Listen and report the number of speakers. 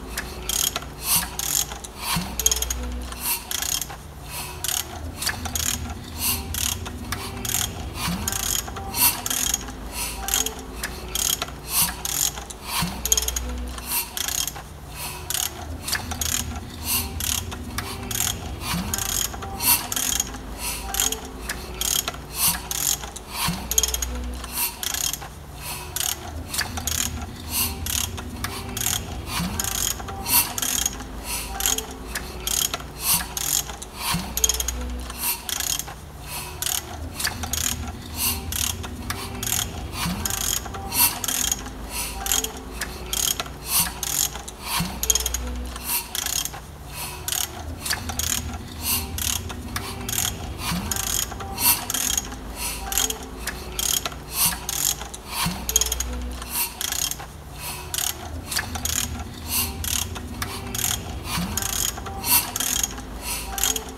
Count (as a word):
zero